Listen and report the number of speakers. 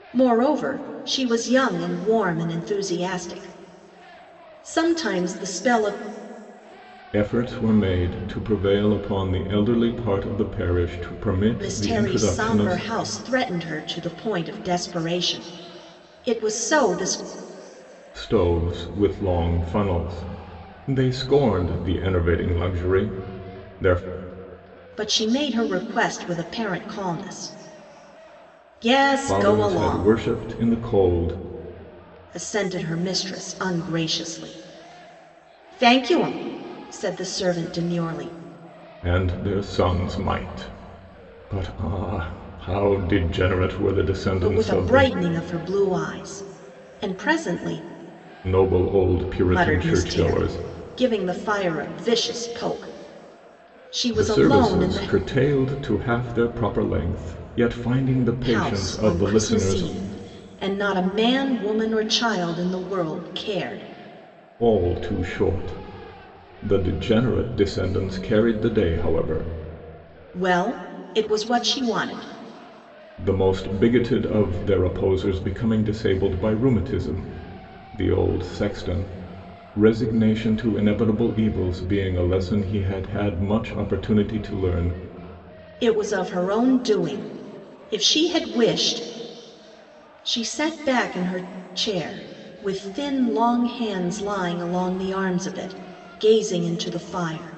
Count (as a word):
two